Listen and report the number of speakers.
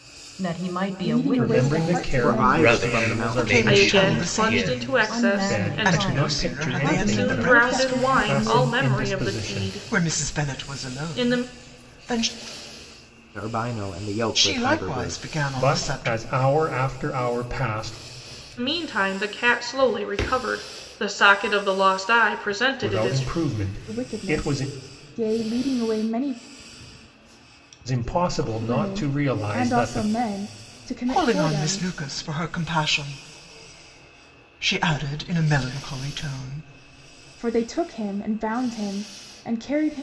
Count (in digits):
7